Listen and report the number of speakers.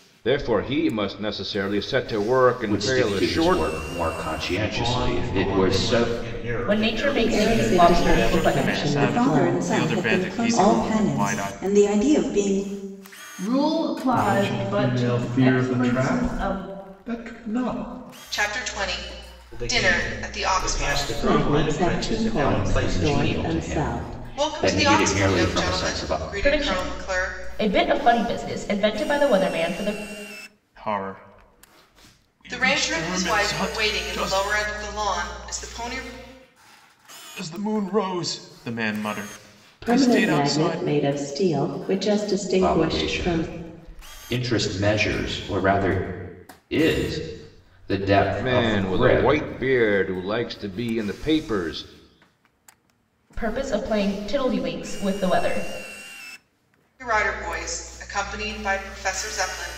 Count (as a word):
ten